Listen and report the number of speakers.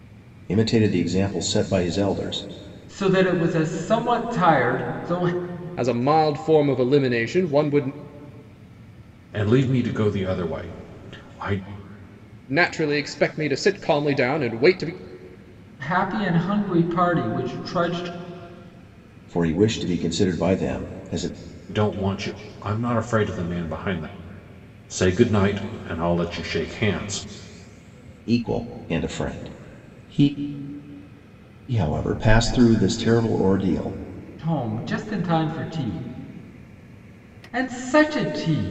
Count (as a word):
four